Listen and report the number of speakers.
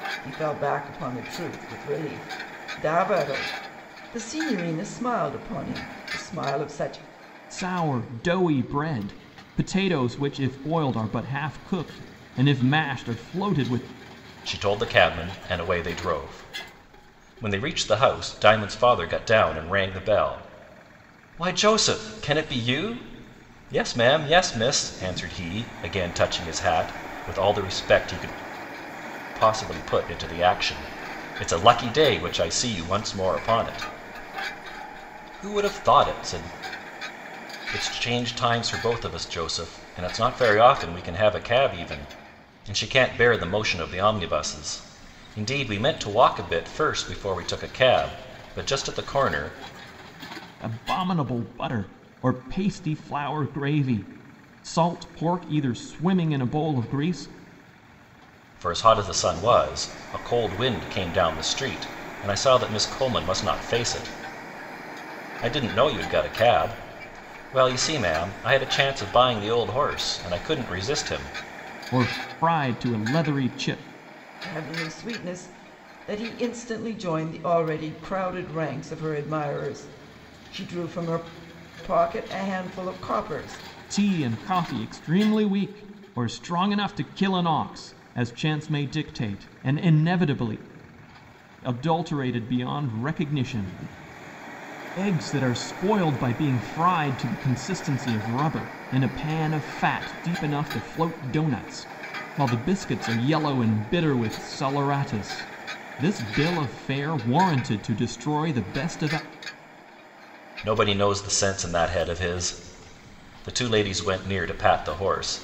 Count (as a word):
three